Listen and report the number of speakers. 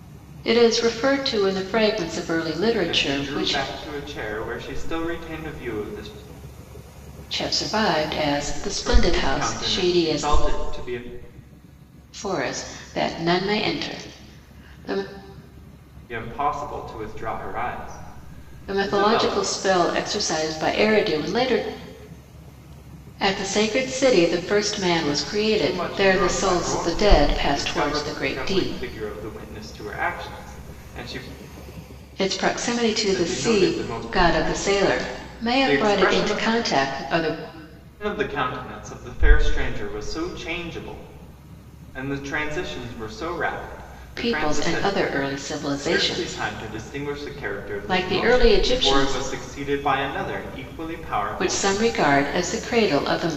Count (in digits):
2